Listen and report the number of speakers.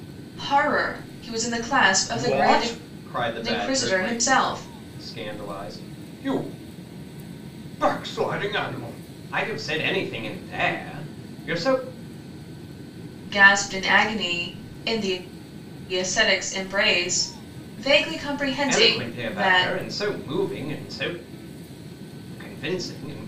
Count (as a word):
two